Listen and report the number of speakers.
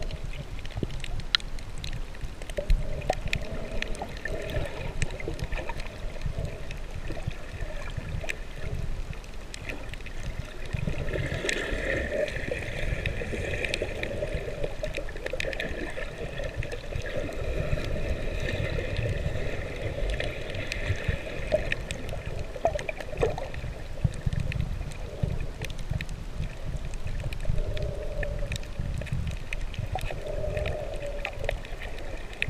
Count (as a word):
zero